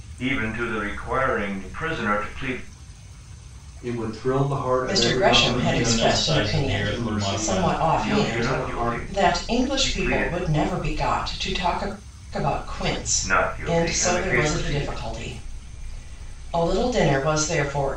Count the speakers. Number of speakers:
four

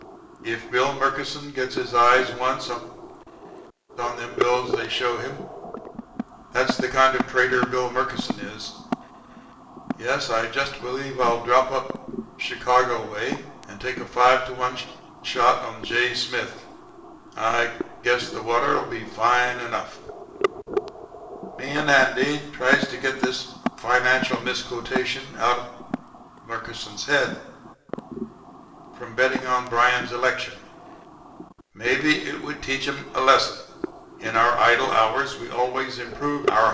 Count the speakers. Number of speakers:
one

